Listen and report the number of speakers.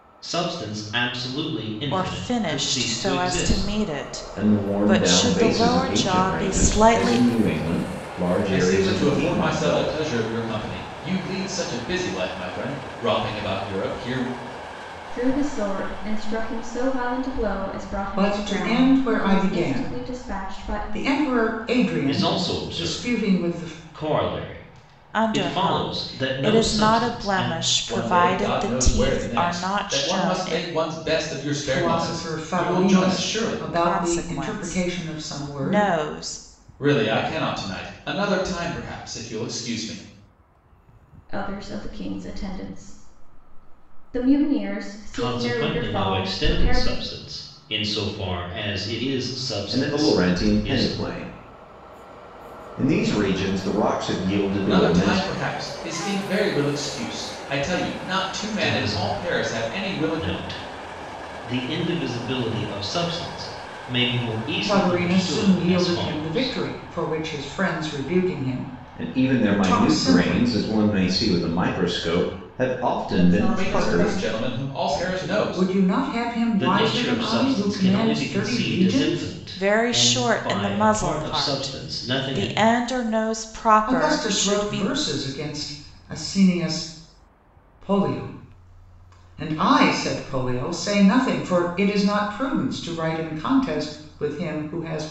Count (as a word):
six